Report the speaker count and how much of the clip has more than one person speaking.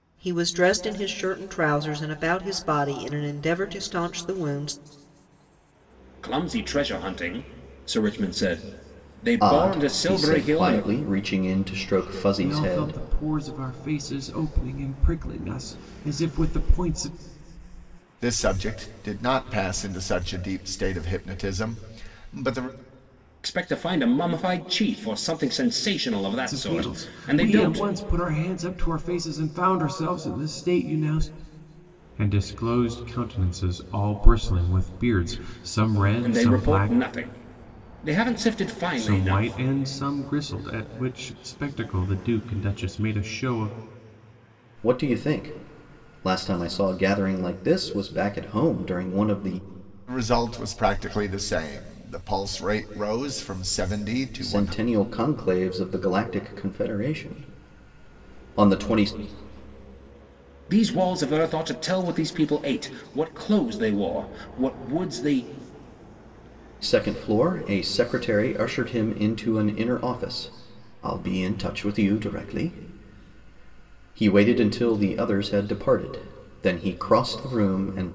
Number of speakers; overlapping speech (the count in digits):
5, about 7%